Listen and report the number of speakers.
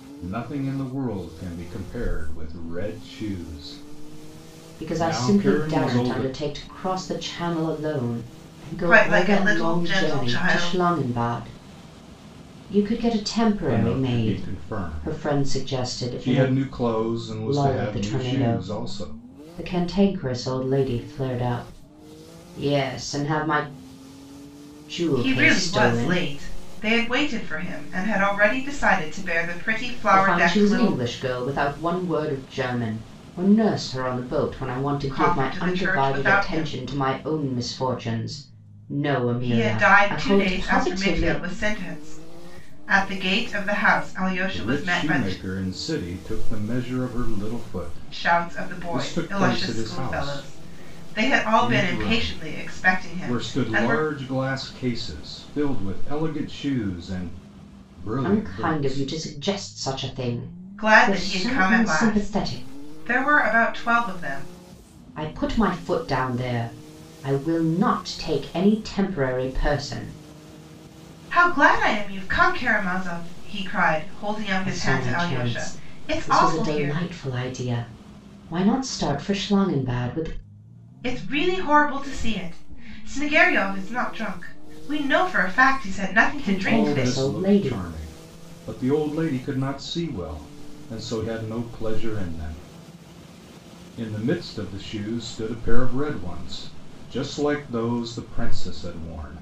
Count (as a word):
three